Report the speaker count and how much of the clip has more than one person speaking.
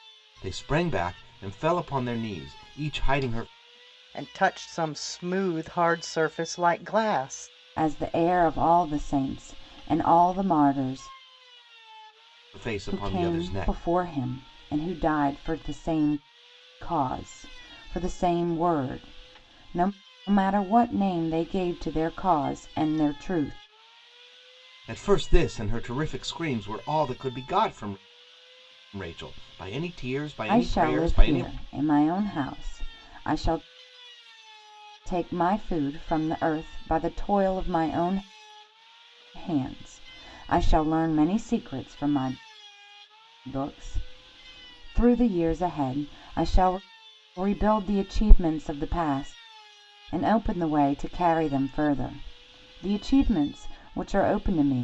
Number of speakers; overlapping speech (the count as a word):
three, about 4%